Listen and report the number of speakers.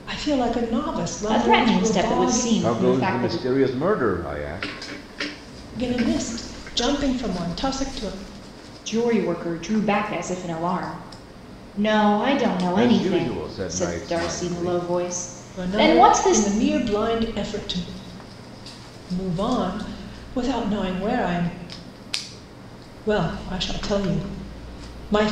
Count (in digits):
3